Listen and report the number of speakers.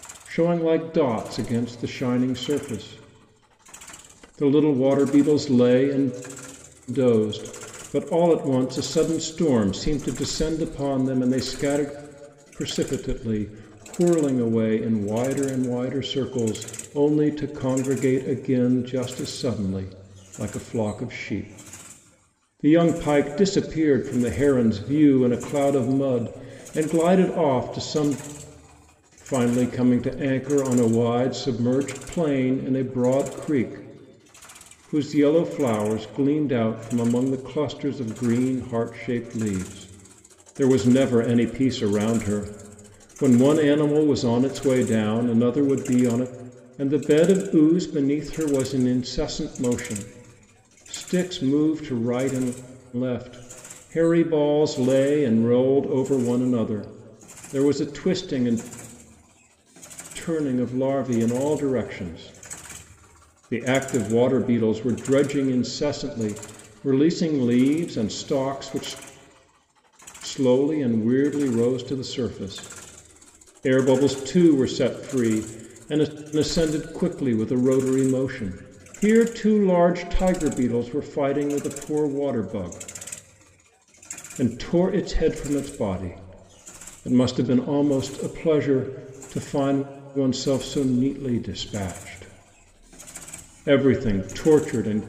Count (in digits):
1